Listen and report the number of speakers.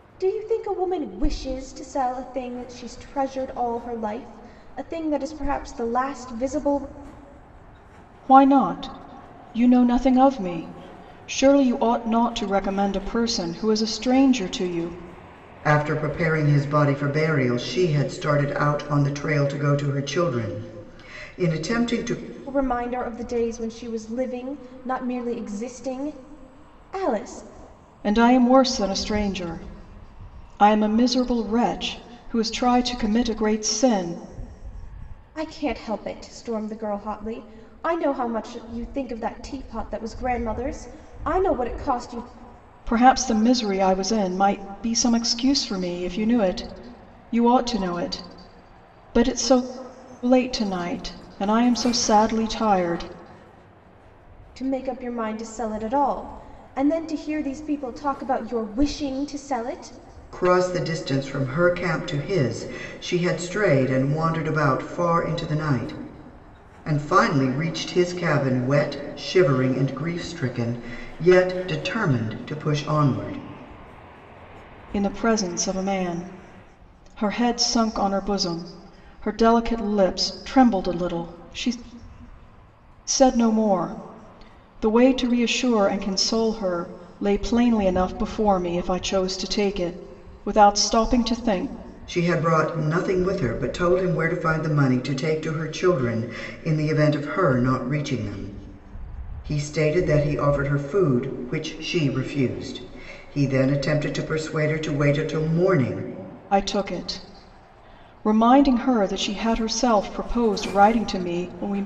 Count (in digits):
3